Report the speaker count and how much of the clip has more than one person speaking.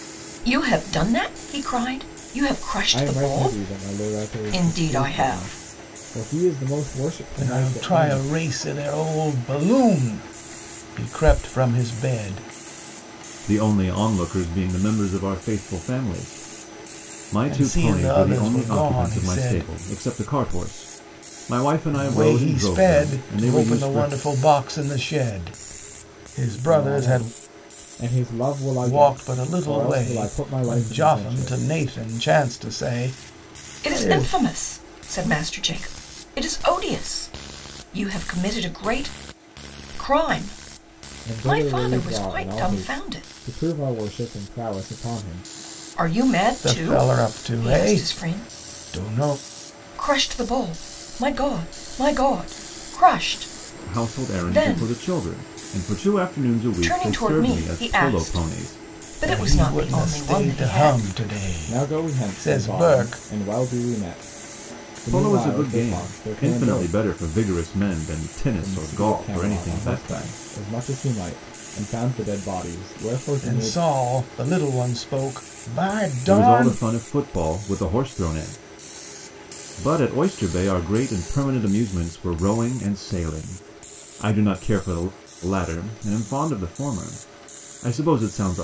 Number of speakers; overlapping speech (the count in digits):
4, about 32%